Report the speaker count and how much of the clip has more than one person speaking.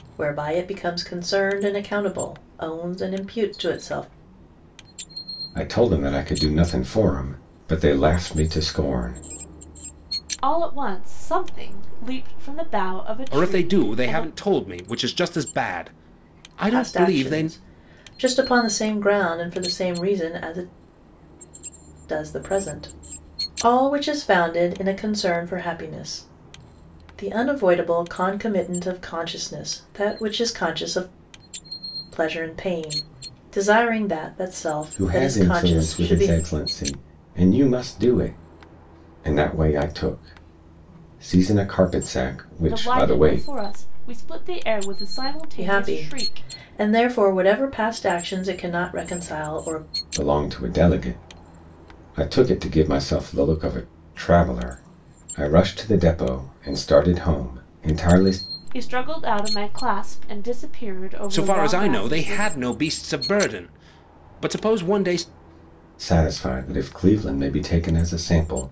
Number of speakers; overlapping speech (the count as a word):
four, about 9%